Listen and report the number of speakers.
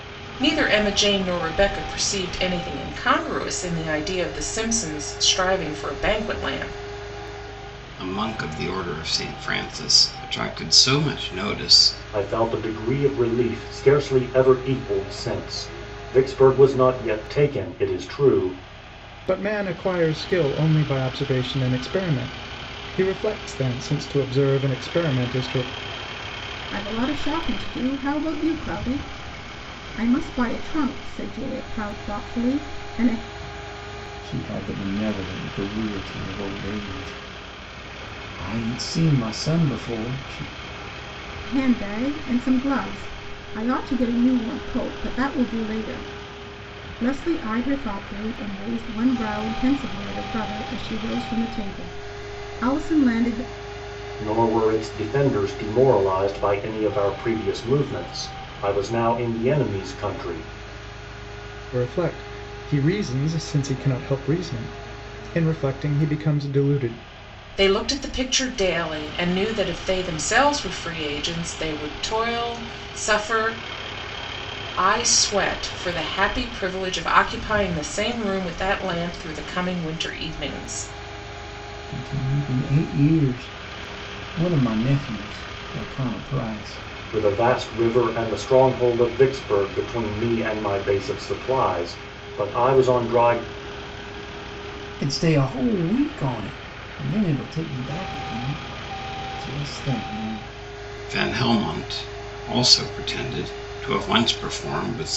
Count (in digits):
6